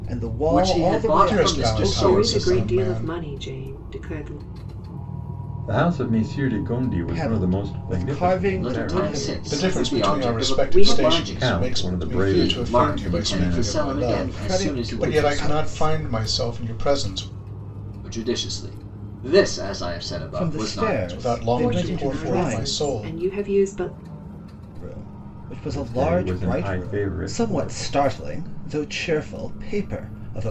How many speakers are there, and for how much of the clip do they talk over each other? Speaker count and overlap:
5, about 54%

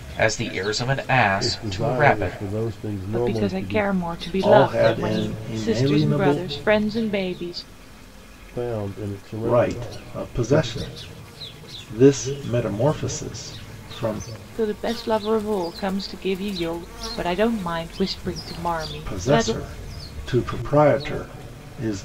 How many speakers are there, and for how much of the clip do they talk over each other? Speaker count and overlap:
4, about 25%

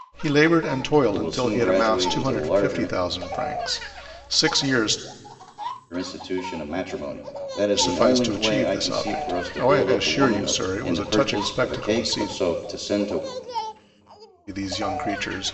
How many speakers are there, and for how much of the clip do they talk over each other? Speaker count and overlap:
2, about 42%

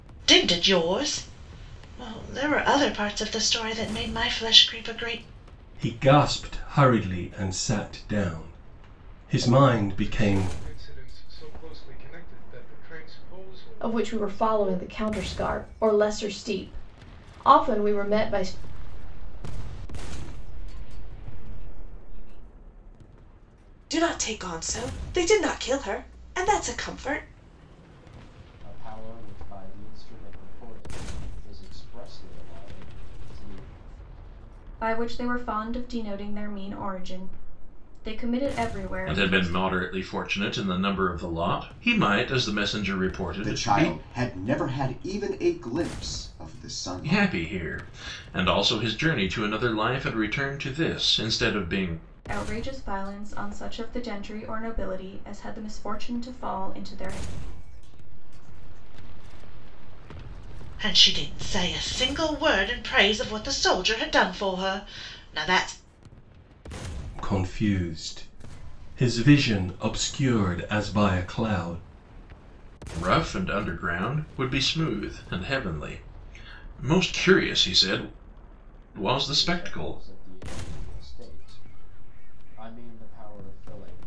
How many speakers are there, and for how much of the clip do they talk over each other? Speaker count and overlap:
10, about 8%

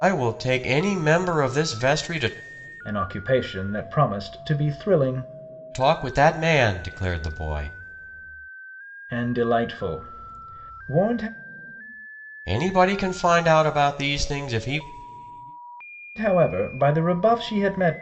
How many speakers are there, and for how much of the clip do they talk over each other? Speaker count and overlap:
2, no overlap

